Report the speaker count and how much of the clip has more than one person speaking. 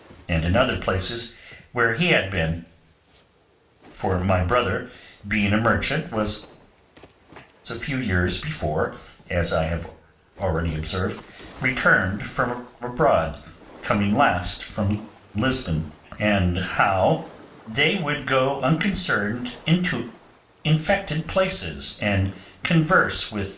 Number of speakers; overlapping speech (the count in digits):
1, no overlap